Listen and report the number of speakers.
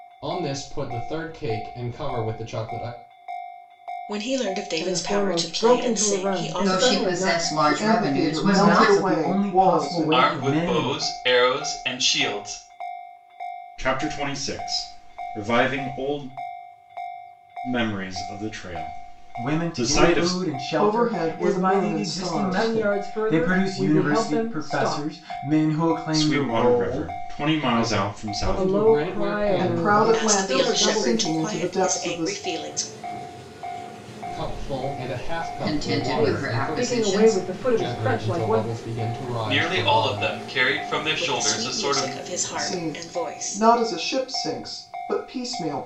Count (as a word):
eight